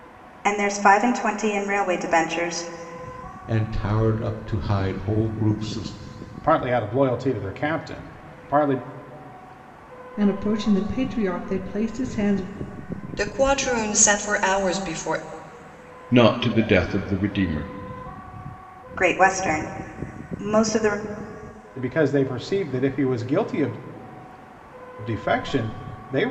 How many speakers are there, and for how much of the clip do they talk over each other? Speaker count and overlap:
six, no overlap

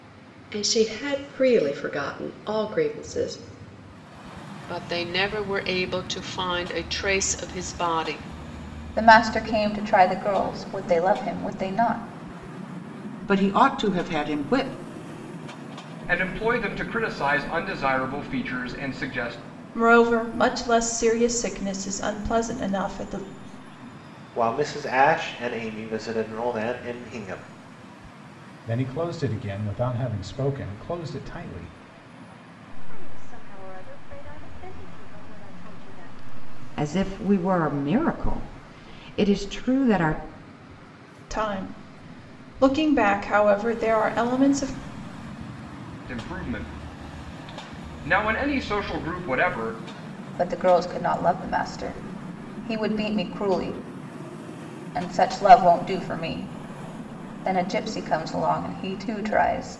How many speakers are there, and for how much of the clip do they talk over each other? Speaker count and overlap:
ten, no overlap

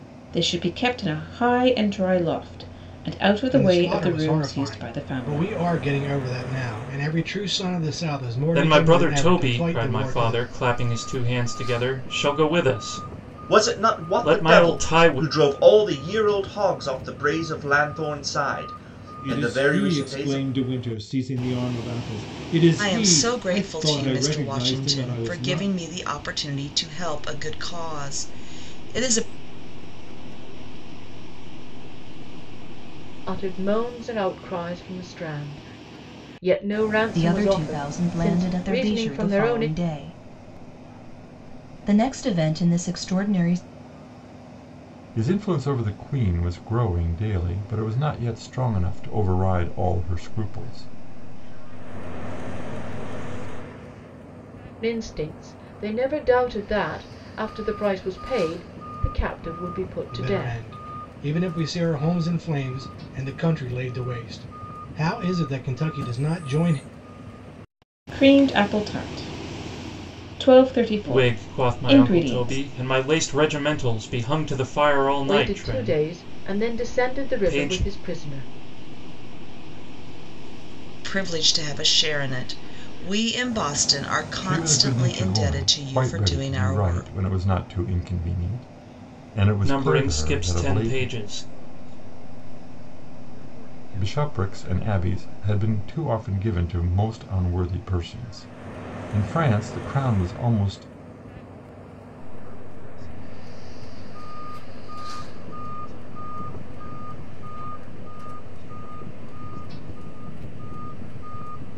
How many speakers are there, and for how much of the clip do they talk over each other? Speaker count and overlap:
ten, about 29%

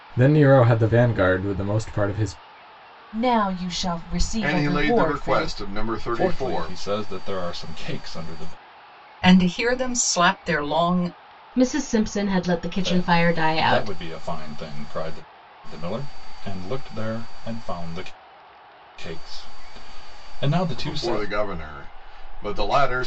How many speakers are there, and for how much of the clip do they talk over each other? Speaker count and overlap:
six, about 16%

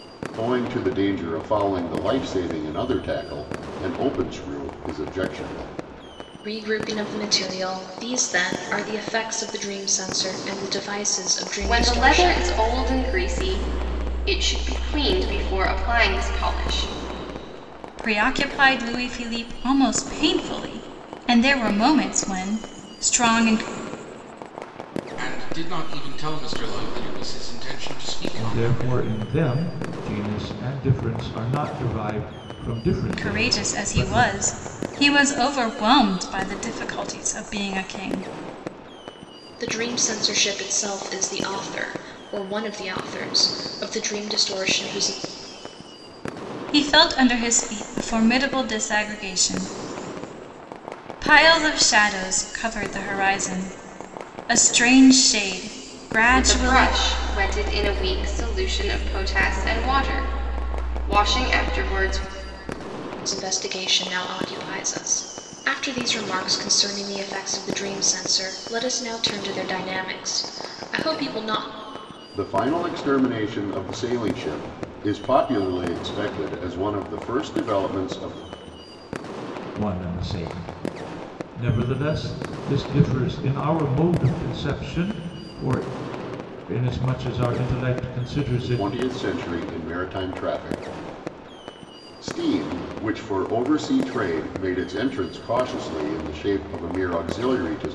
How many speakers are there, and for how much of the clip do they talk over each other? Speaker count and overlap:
six, about 4%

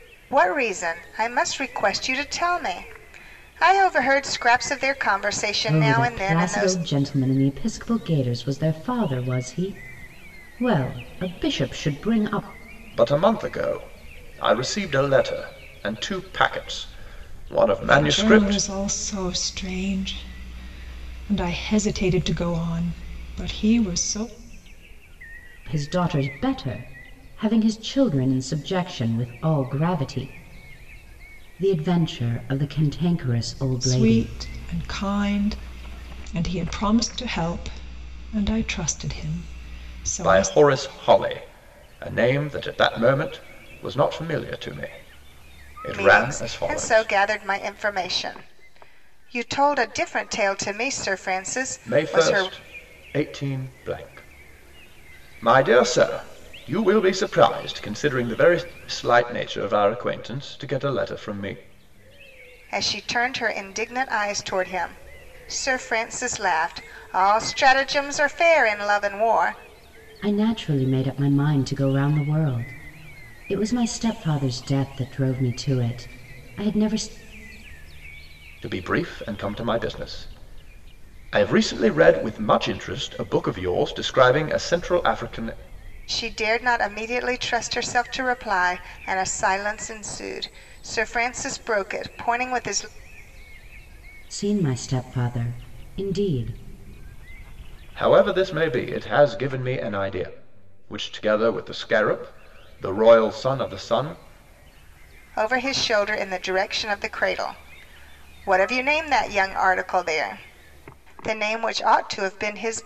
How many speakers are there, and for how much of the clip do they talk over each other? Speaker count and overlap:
four, about 4%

